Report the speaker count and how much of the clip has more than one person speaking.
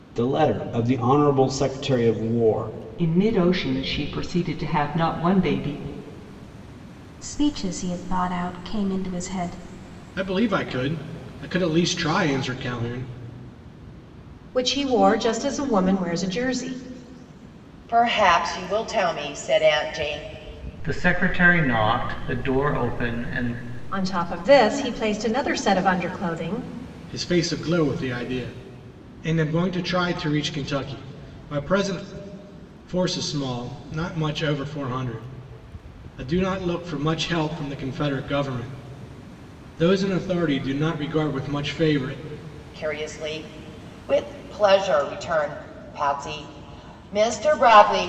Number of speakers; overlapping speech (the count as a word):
seven, no overlap